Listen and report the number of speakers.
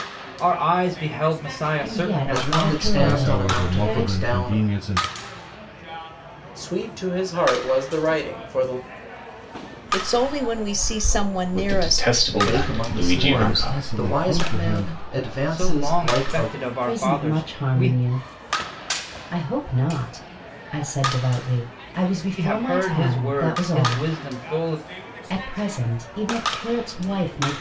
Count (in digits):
7